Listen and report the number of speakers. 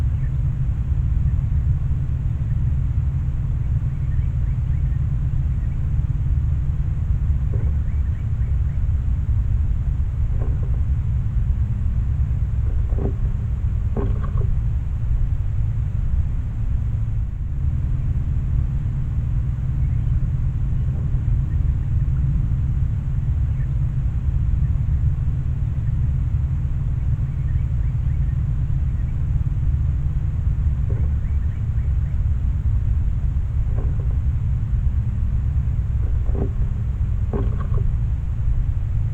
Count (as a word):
zero